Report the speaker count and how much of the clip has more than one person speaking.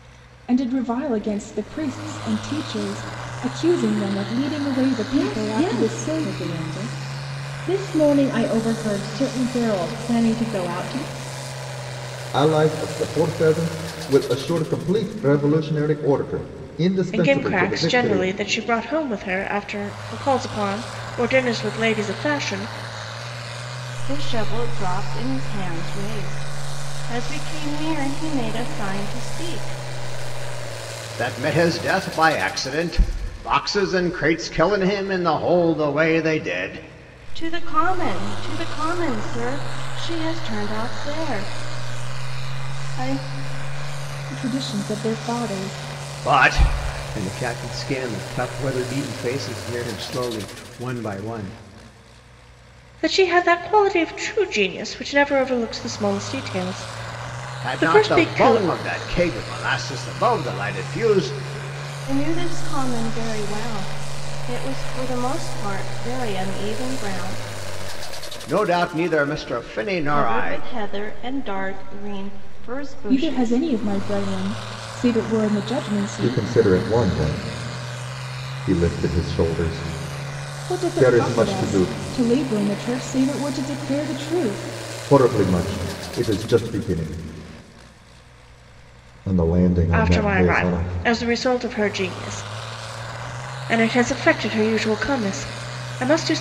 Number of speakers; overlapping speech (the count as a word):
six, about 8%